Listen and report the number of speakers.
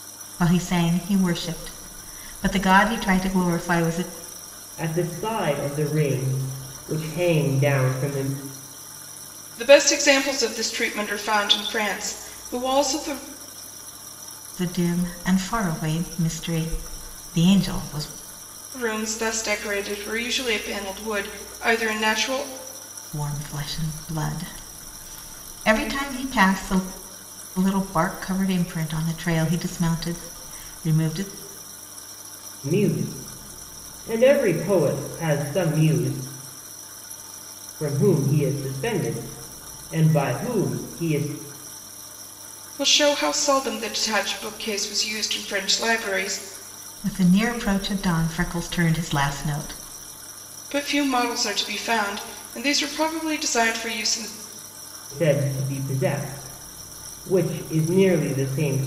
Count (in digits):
3